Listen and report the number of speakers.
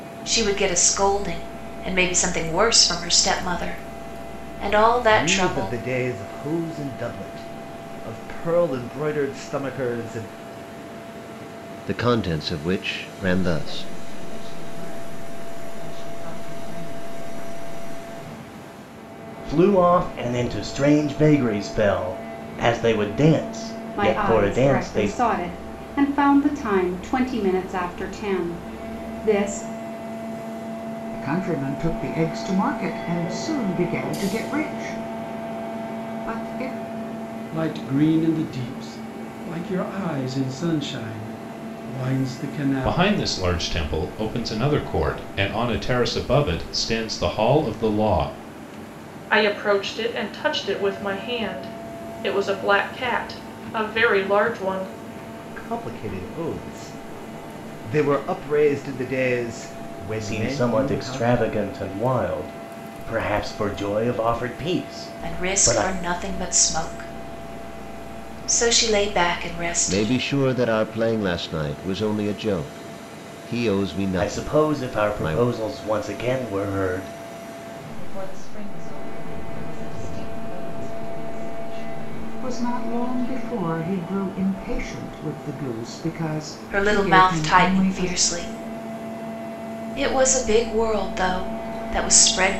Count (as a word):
ten